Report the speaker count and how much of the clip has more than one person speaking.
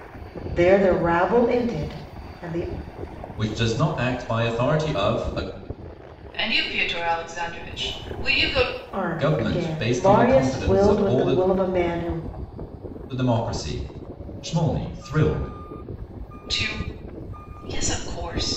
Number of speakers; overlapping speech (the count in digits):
3, about 12%